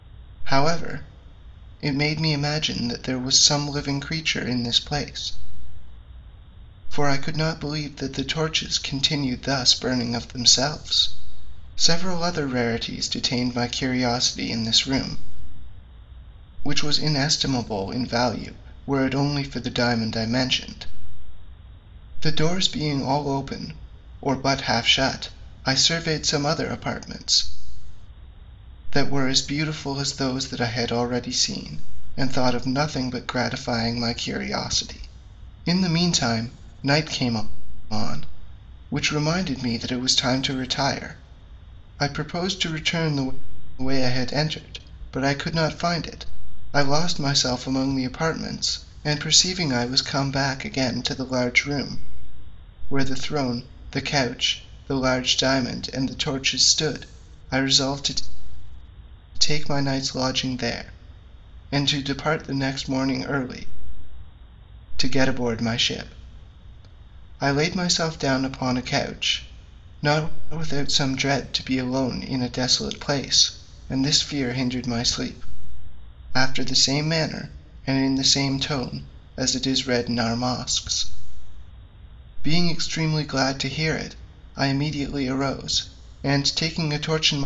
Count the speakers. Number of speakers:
1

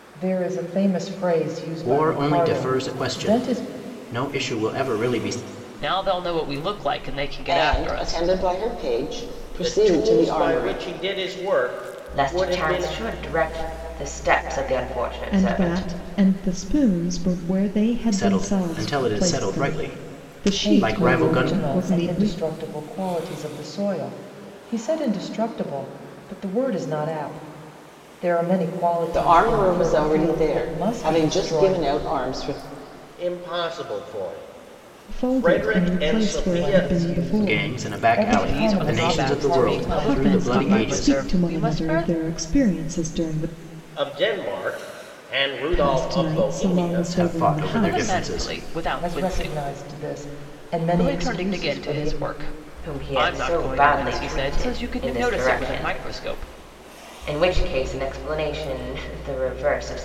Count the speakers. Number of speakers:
7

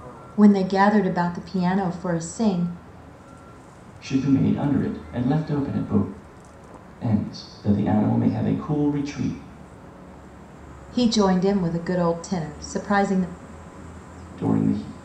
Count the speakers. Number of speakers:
2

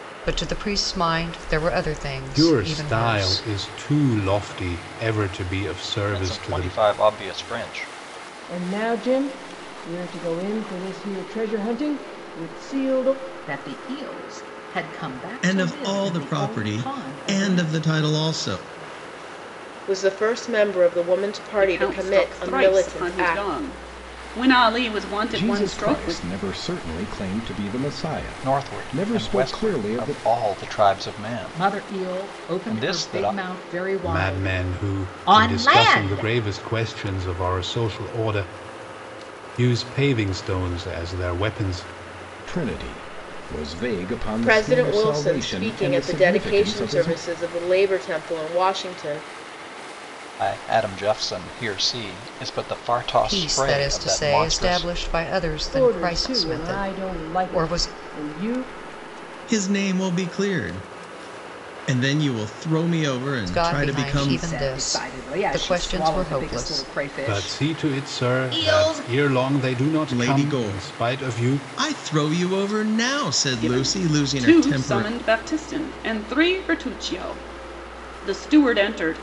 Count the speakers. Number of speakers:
9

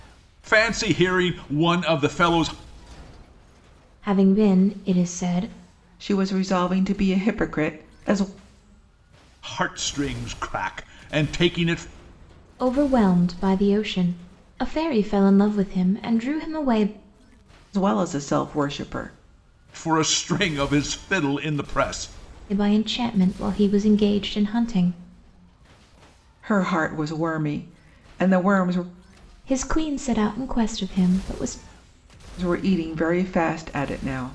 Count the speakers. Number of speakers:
3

